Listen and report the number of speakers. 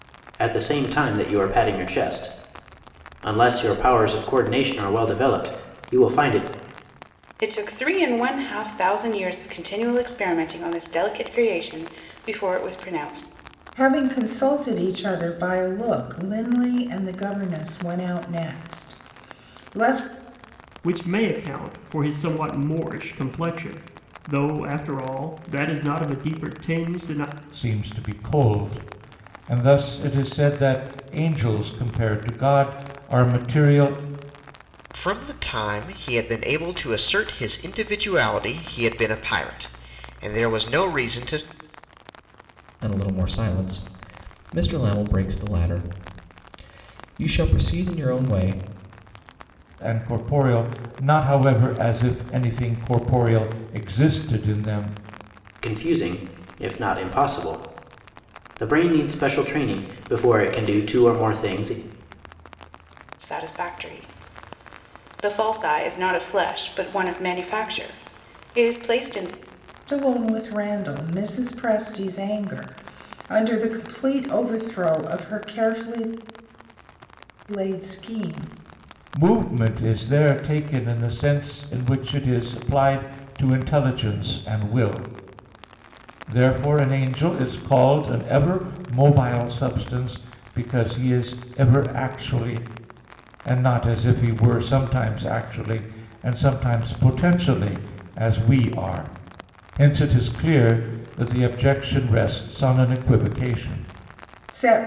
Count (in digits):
7